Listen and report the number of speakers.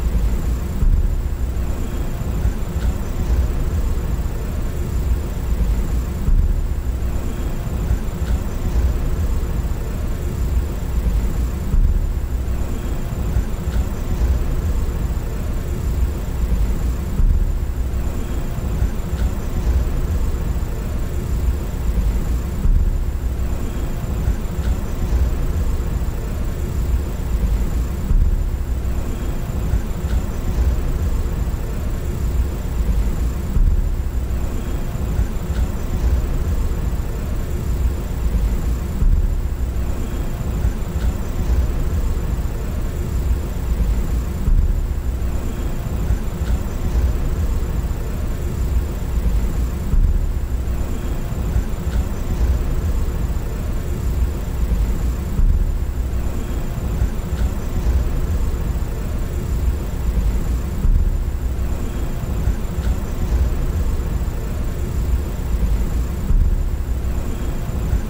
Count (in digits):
0